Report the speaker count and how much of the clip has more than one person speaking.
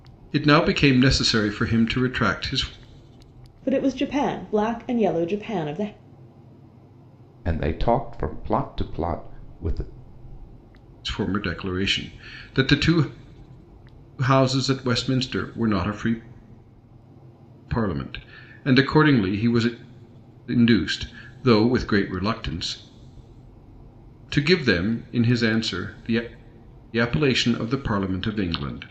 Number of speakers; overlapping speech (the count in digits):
3, no overlap